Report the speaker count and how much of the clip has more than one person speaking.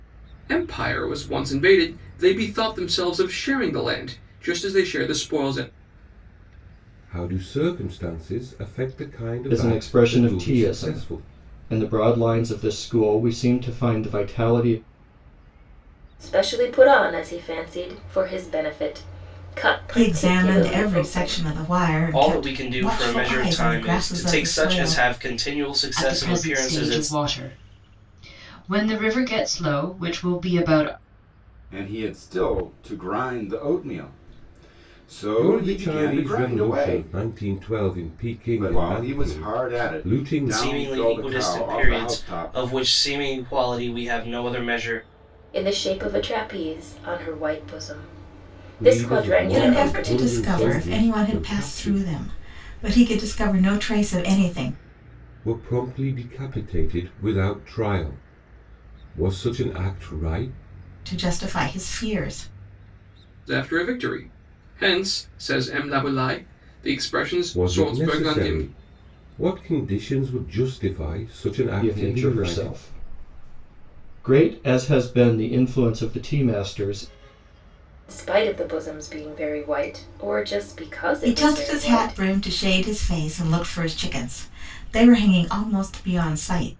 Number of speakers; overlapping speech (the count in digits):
8, about 23%